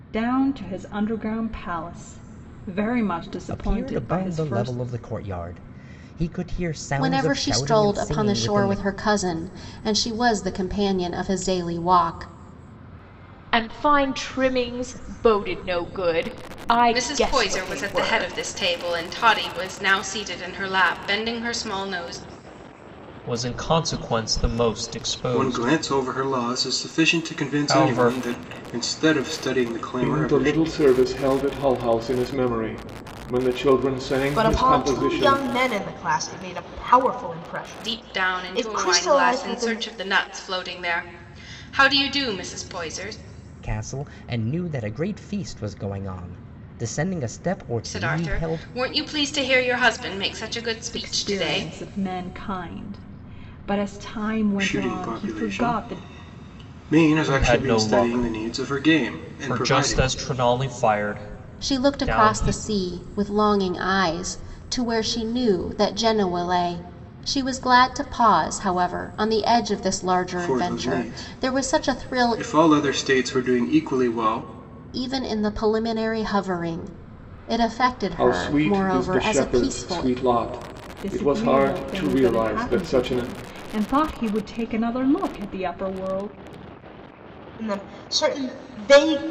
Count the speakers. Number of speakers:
nine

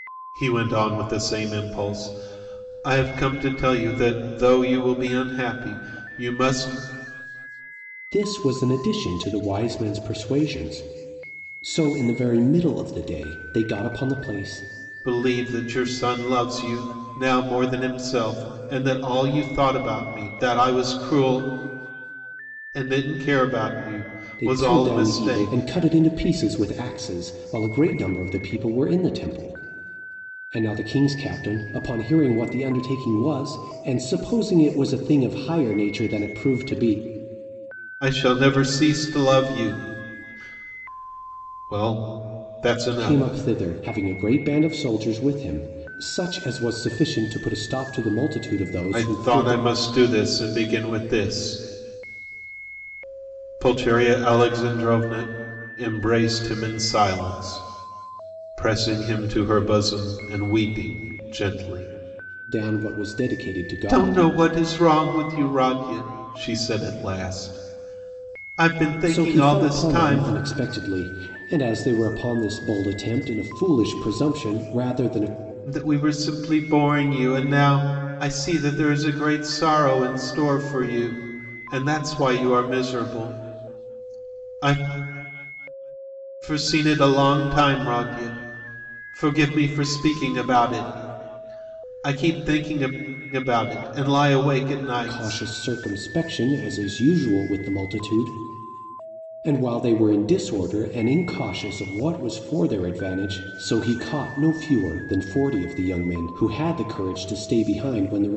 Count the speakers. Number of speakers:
two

